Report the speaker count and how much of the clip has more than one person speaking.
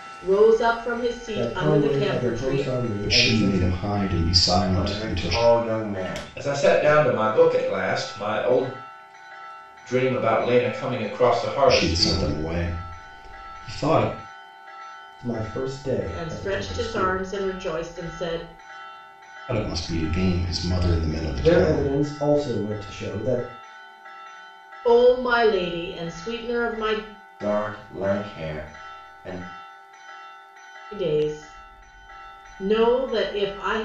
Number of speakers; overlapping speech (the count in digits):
5, about 18%